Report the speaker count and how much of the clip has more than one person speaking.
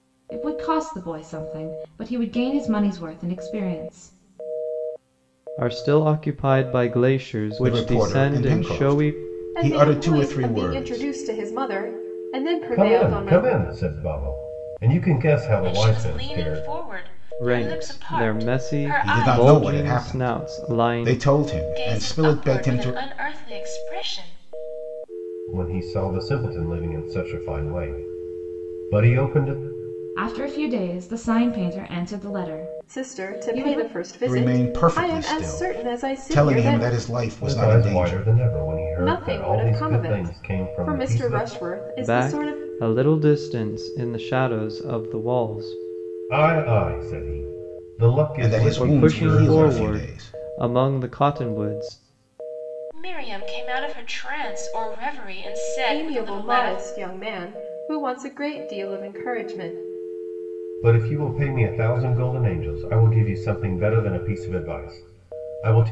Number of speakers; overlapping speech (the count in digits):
6, about 32%